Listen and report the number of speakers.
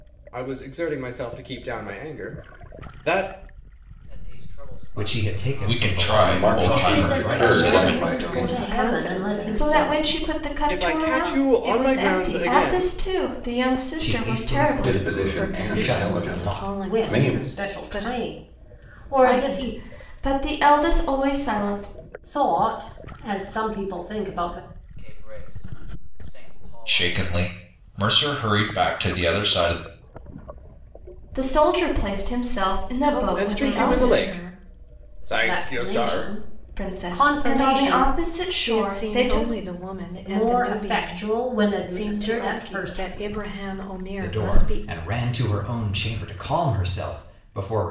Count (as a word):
eight